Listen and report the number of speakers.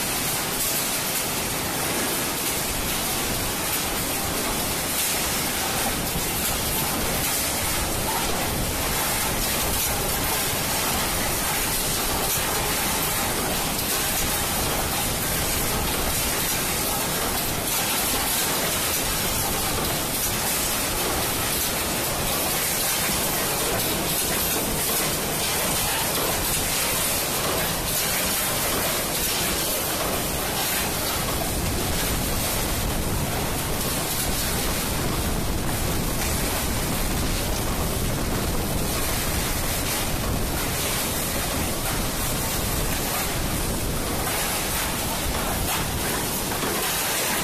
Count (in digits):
0